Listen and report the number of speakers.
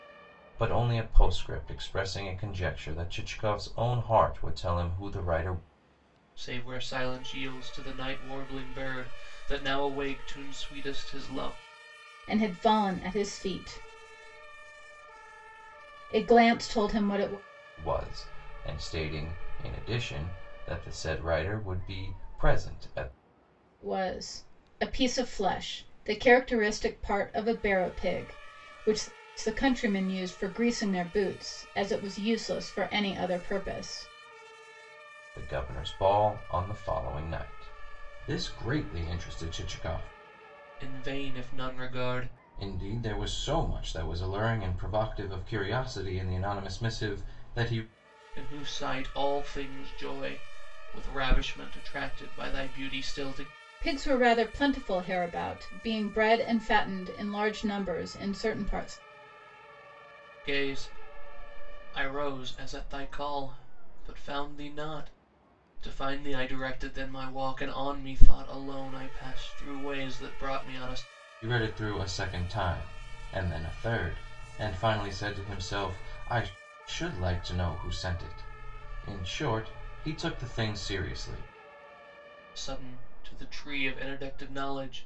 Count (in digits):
3